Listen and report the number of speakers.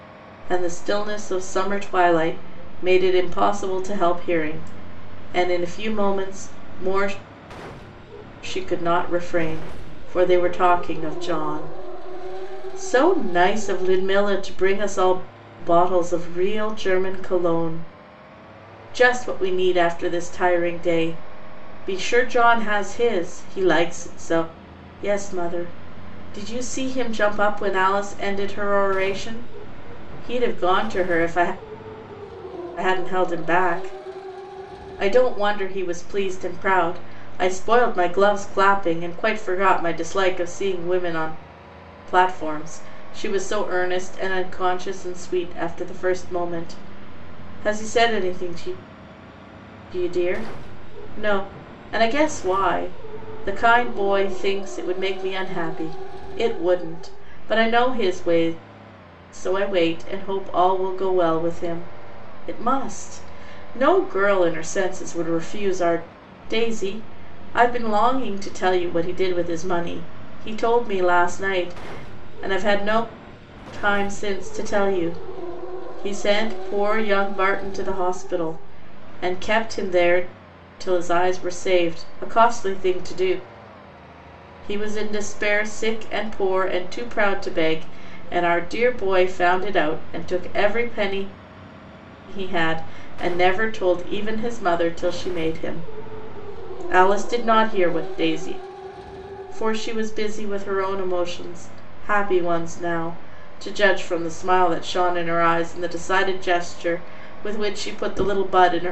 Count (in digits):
1